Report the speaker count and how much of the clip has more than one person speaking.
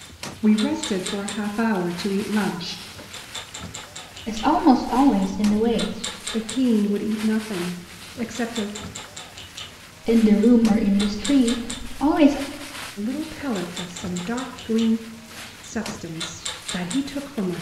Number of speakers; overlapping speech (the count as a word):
two, no overlap